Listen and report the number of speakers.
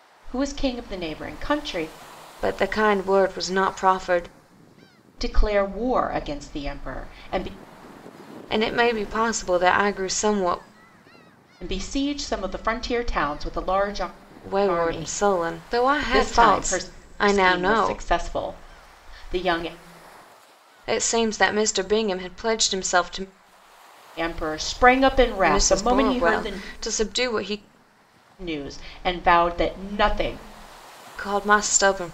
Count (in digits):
2